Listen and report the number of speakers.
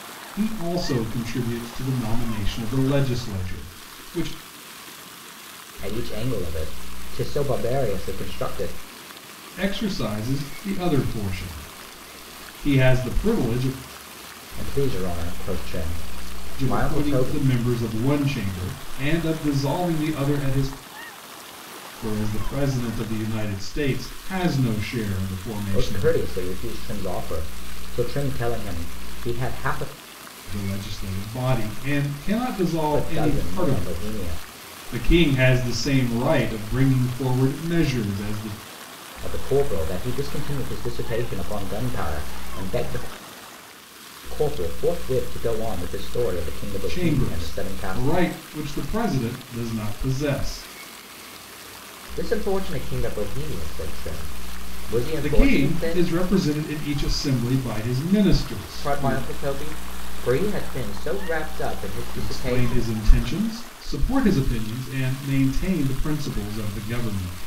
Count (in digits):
2